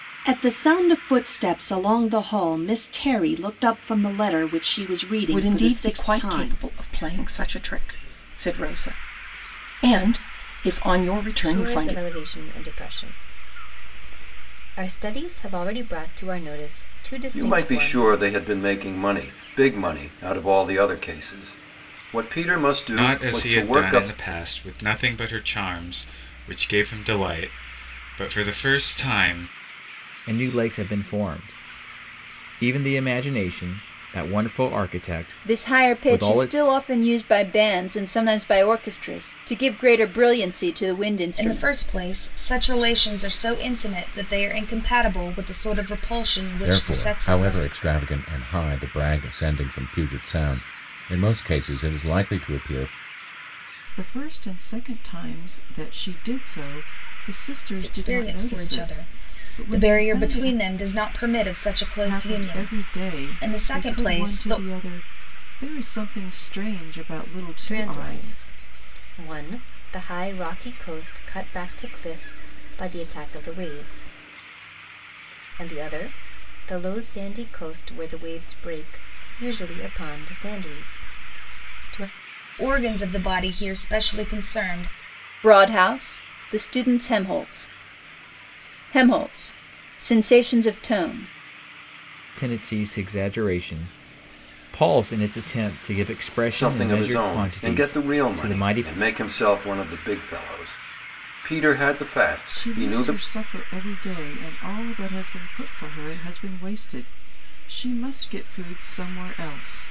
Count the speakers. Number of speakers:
10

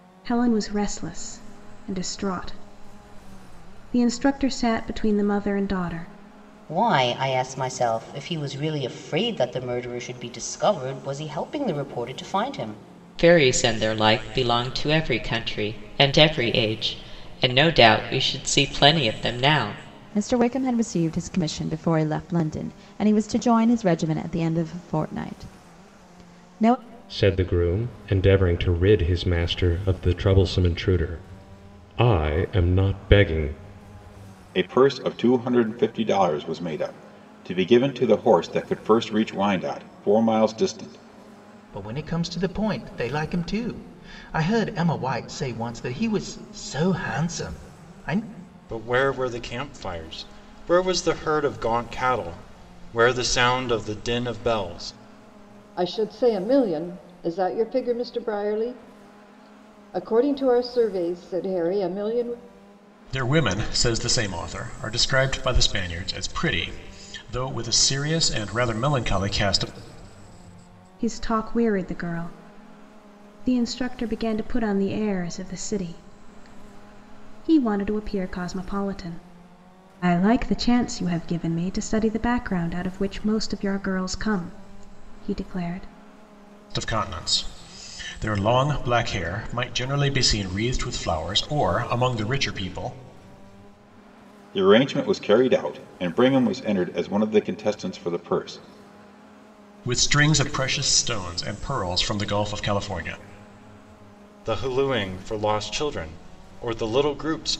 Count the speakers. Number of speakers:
10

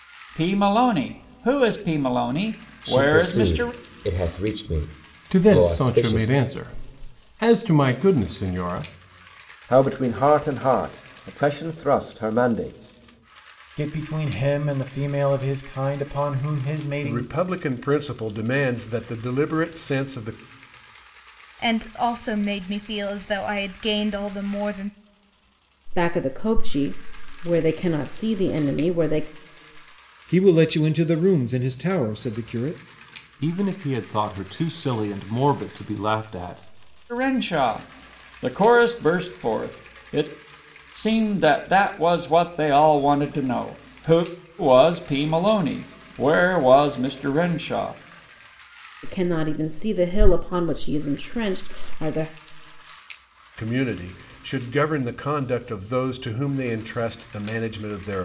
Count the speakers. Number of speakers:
10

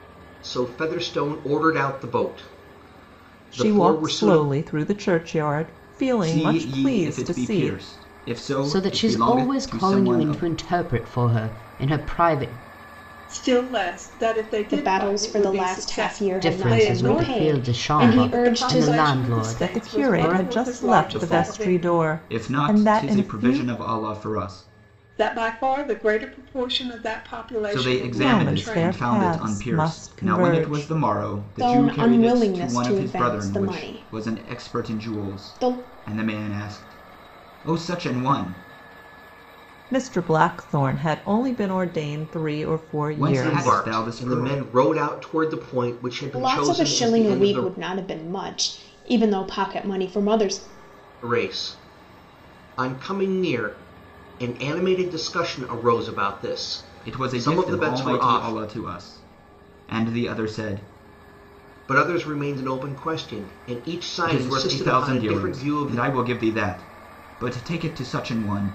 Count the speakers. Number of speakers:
6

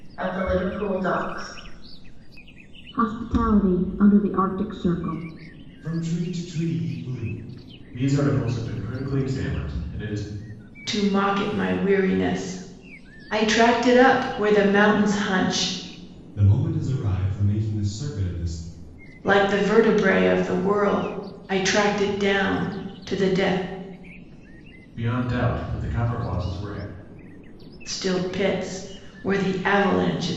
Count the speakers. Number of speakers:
5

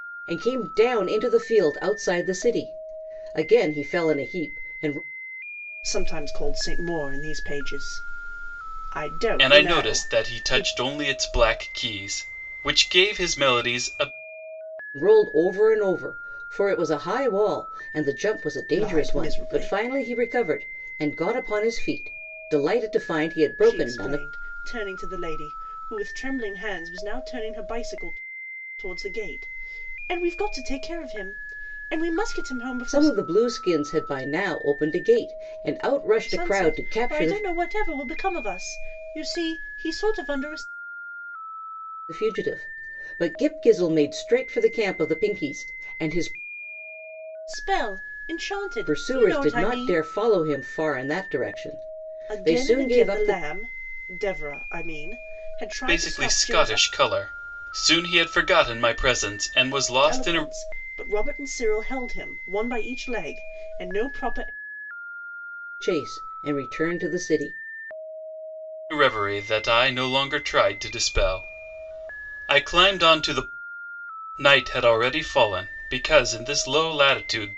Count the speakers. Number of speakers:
3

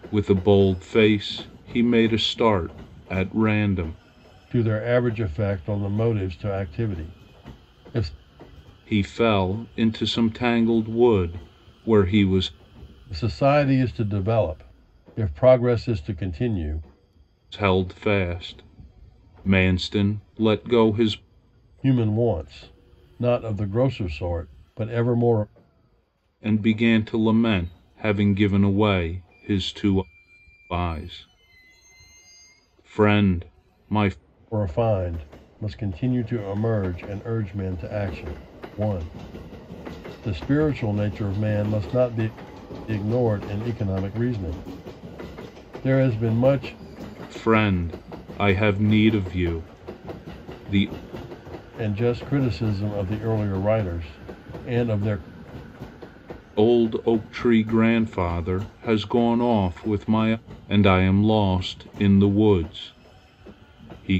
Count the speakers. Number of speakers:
2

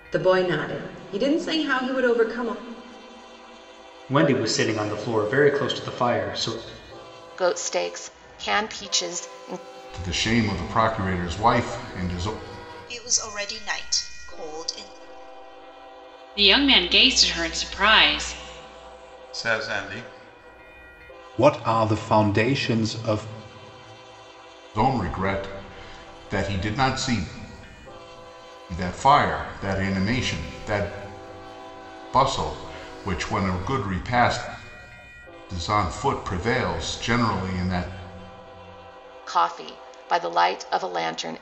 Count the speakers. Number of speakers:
8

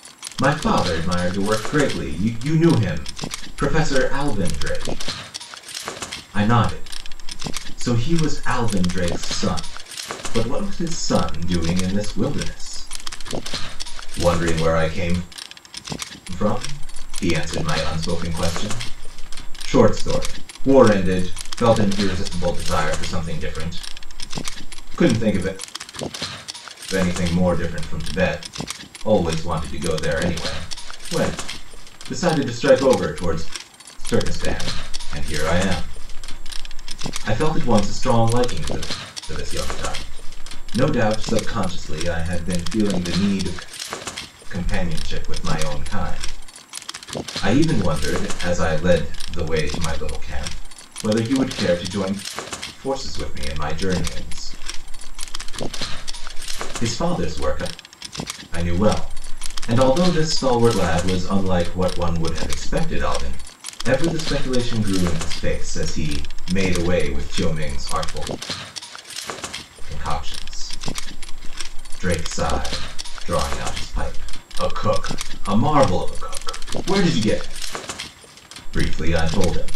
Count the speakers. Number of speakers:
1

